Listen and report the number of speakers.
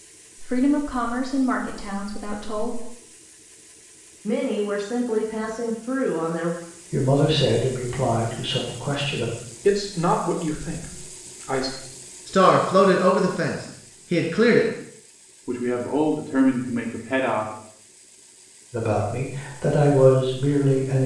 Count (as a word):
six